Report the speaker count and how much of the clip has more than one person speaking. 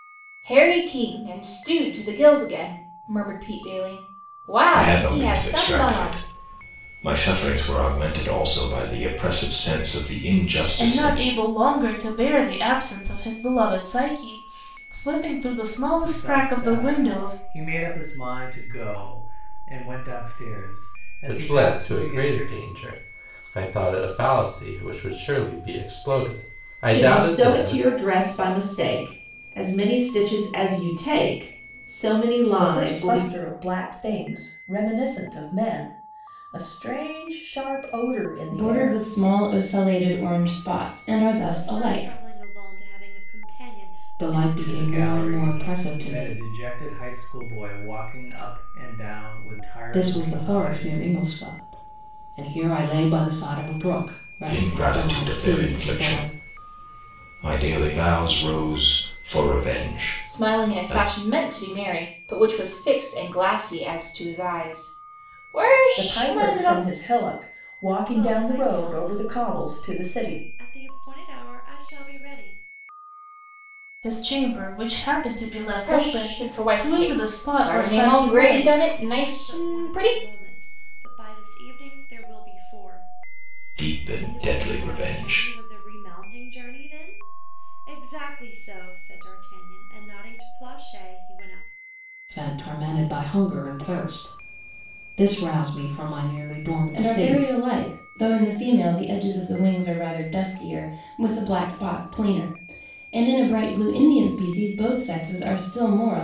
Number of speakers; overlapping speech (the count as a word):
ten, about 23%